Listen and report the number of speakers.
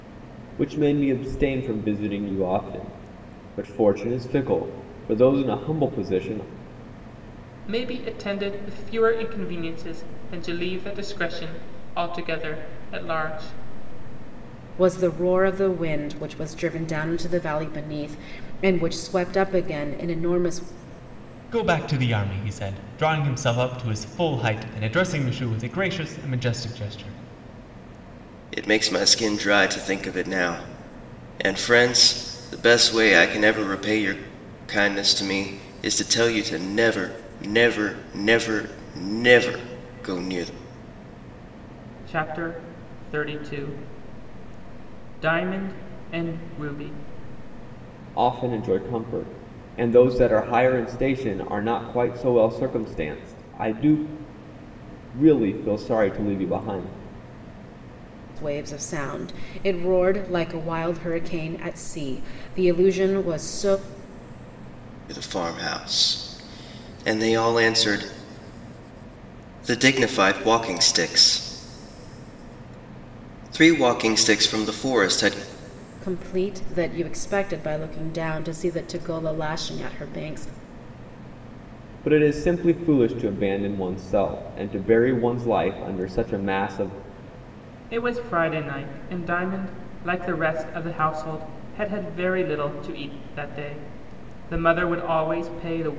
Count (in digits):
5